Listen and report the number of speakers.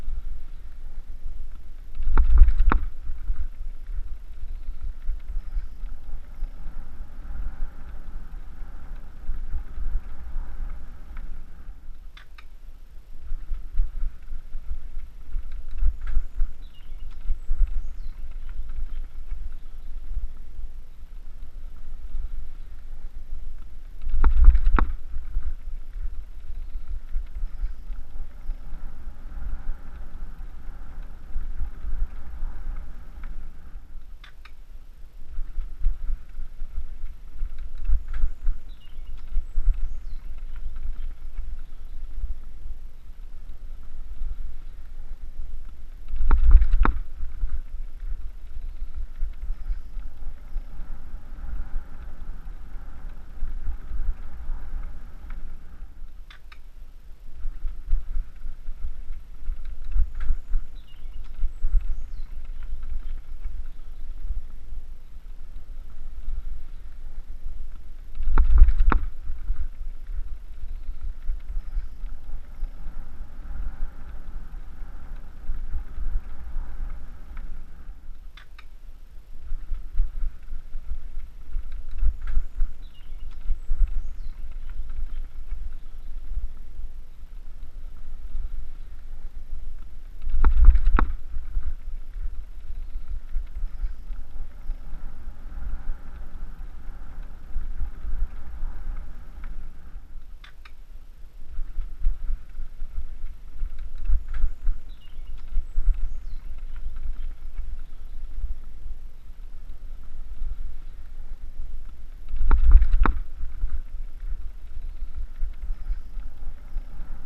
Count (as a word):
zero